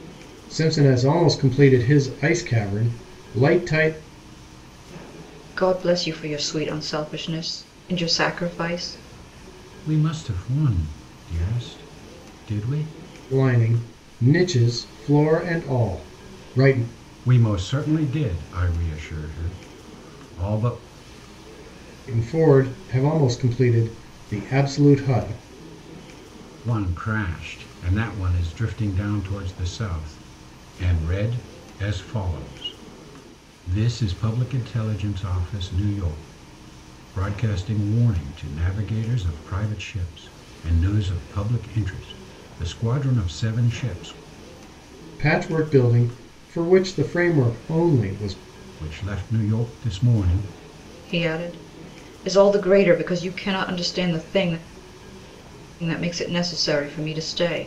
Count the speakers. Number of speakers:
three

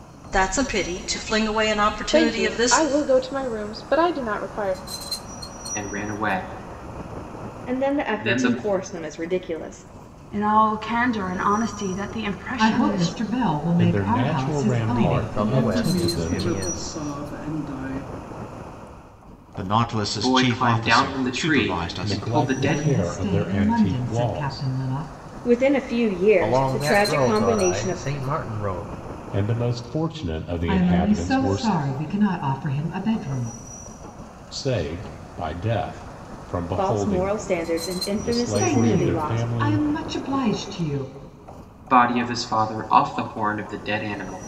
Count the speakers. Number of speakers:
ten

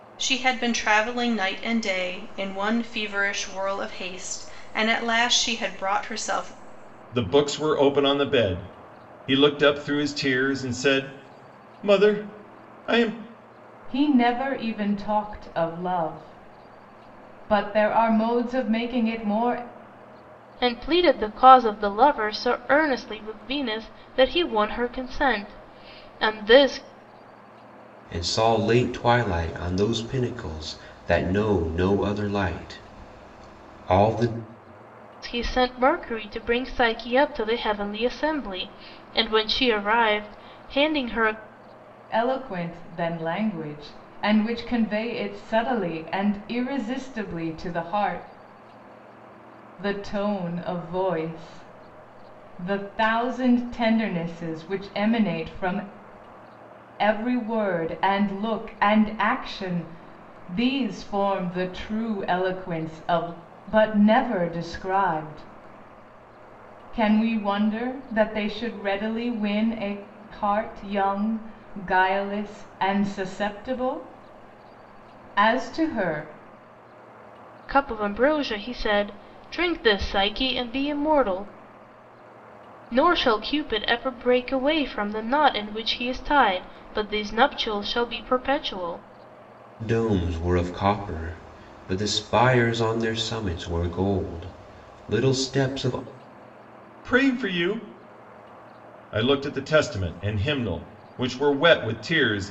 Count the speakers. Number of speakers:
five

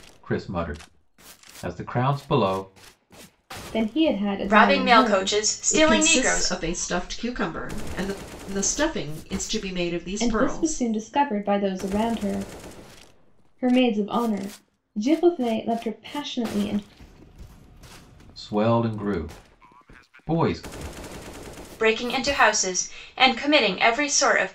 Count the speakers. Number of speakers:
four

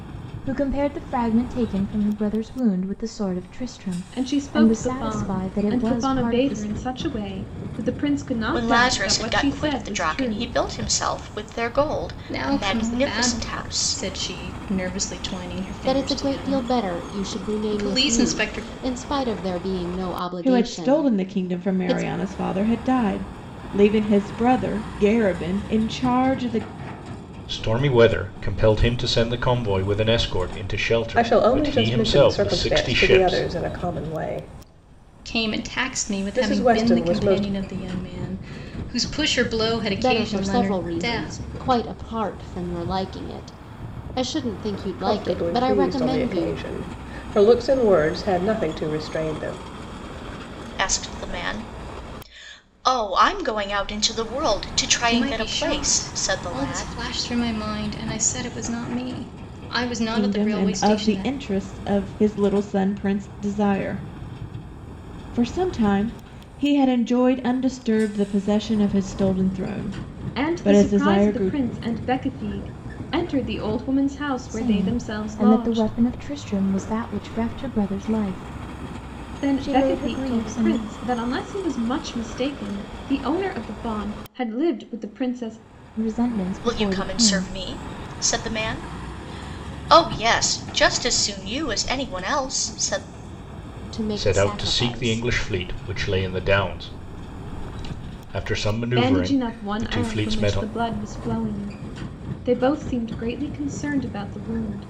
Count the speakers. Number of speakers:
eight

